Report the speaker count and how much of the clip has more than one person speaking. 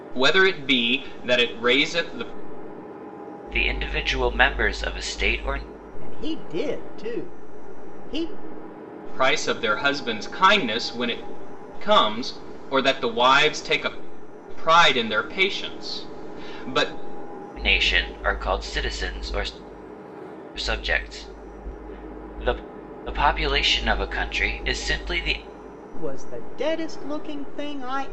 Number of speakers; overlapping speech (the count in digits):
3, no overlap